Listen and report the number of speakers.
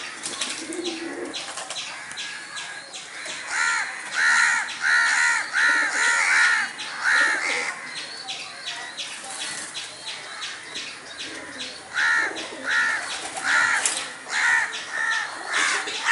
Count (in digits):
0